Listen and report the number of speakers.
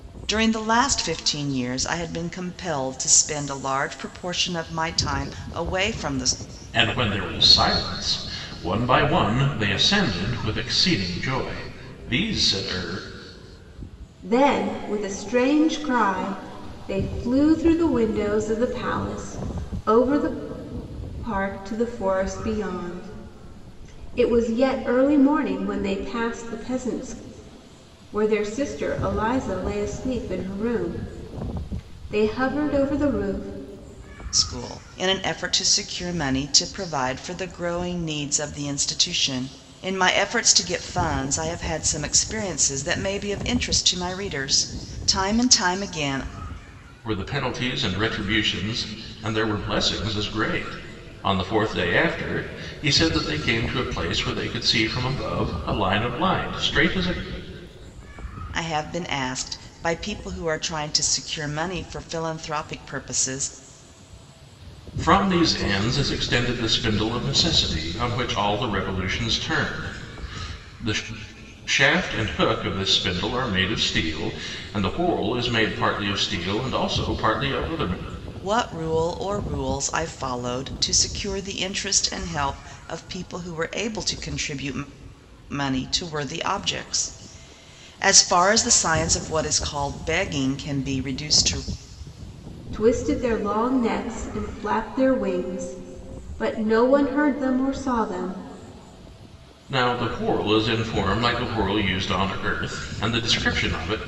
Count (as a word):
three